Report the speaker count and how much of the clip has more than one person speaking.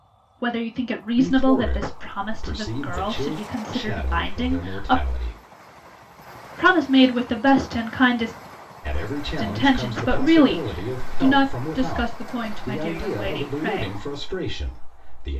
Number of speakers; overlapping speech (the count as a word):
two, about 52%